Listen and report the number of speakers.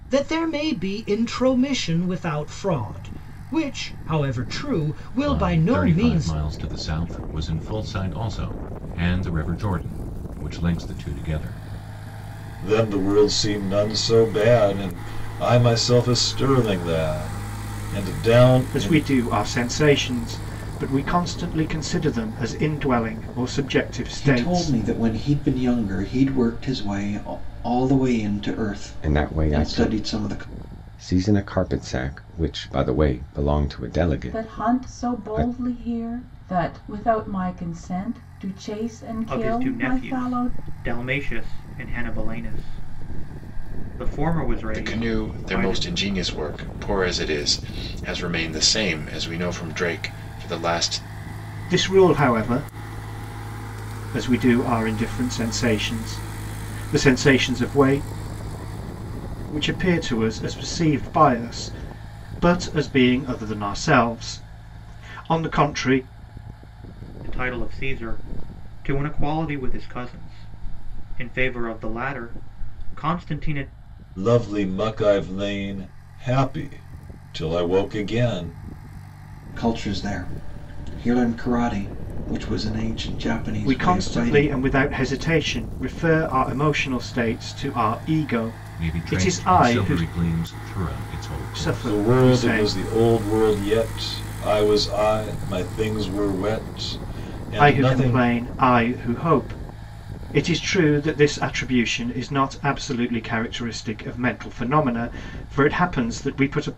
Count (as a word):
nine